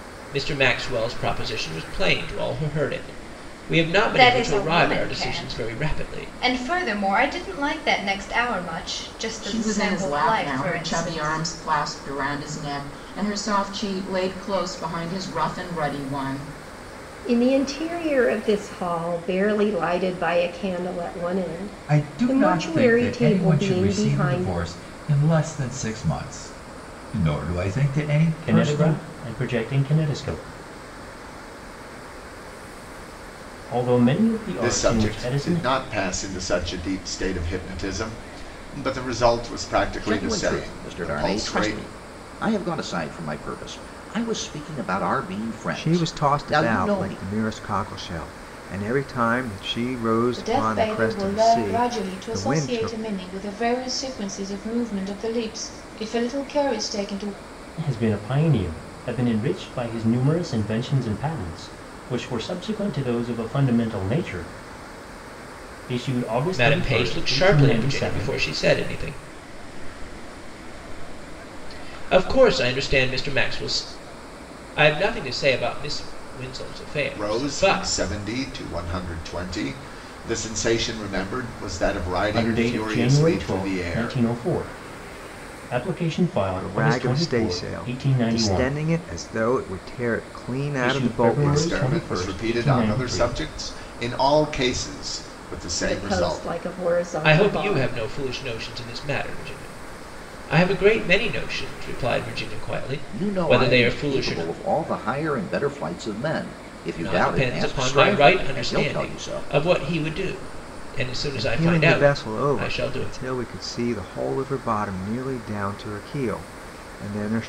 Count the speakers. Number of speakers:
10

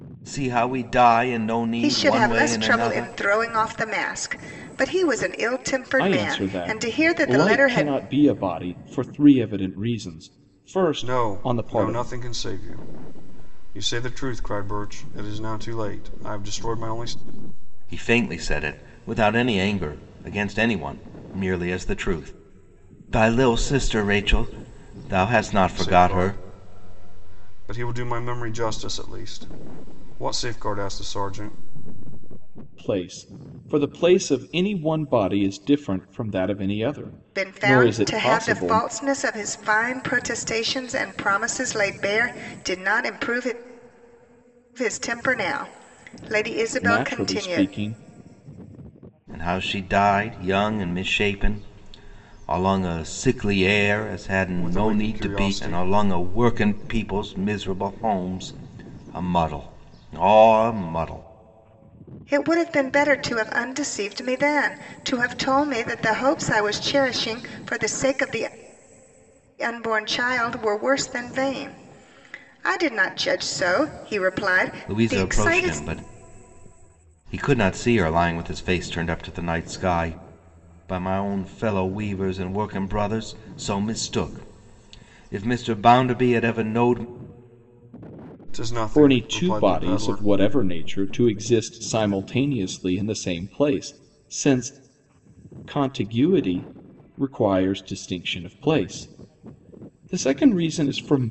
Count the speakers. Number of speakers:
4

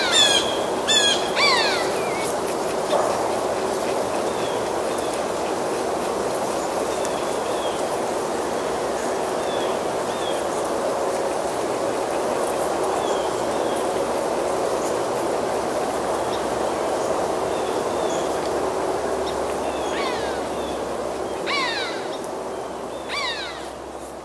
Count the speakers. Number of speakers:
0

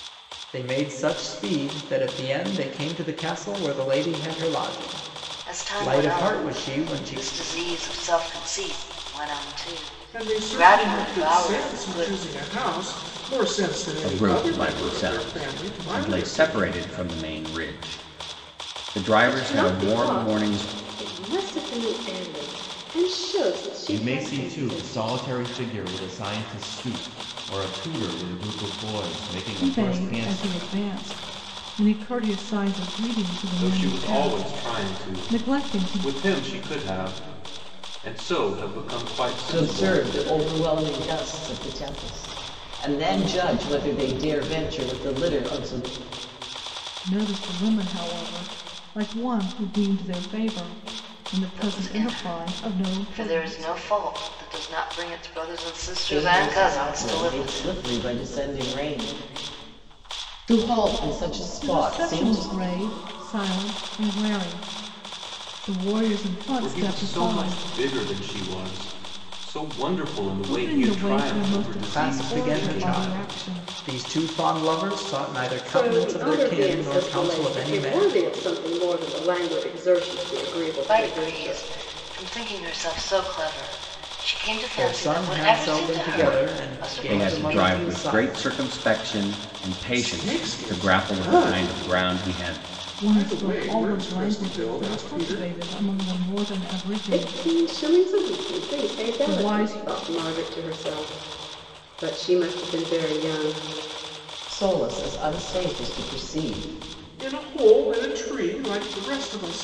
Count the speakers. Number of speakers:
9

